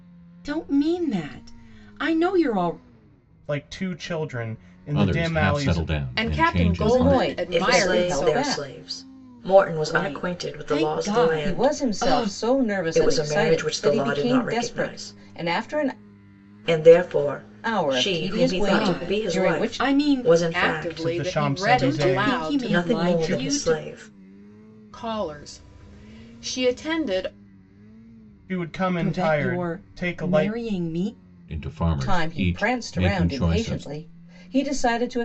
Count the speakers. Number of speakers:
6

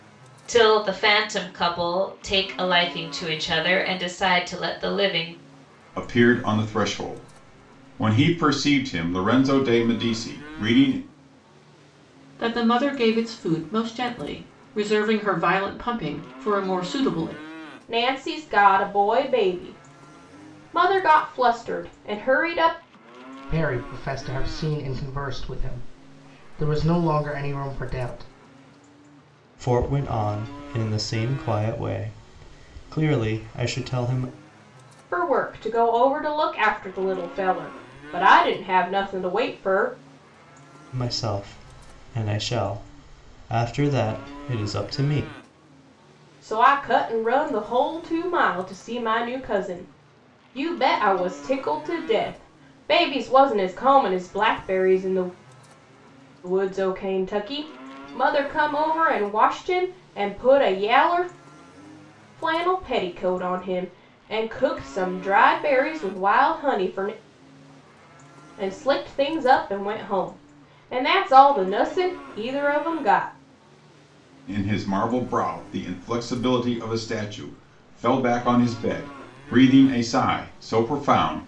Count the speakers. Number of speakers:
6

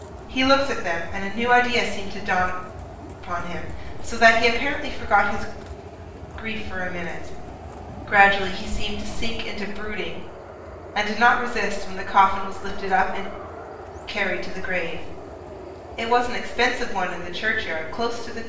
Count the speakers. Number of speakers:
1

